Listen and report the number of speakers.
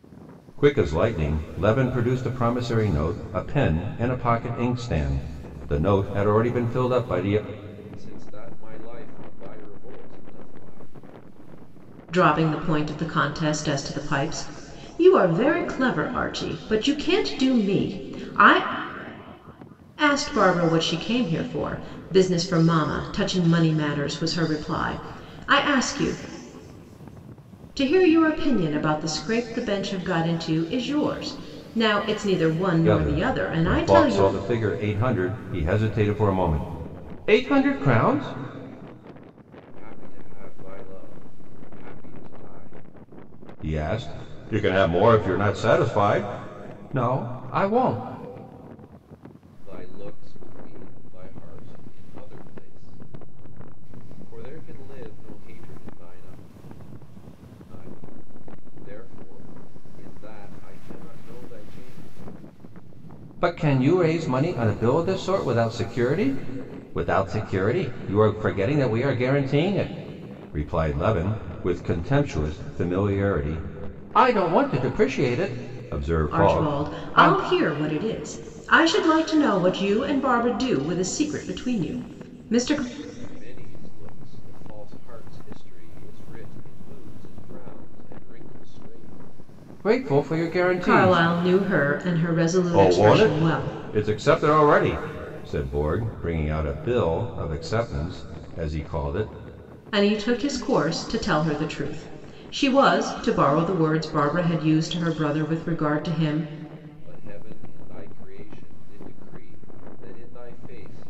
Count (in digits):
3